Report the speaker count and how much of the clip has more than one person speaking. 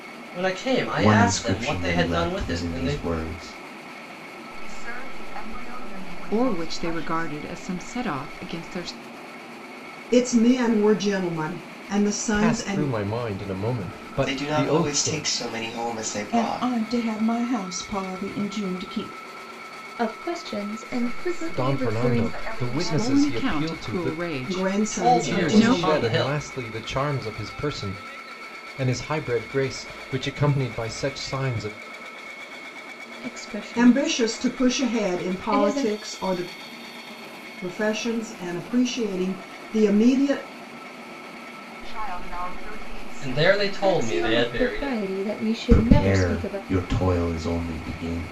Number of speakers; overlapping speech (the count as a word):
nine, about 33%